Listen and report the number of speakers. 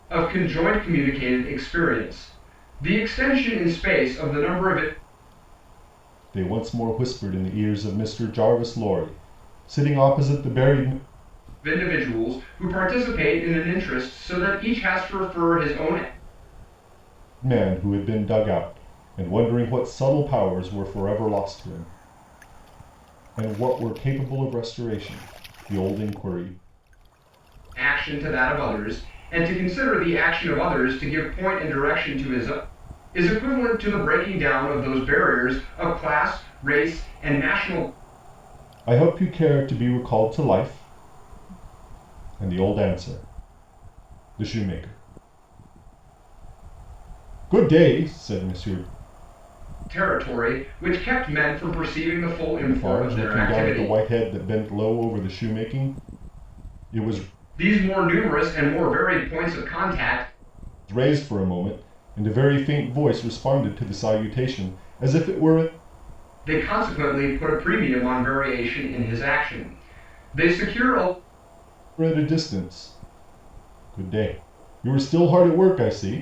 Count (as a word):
two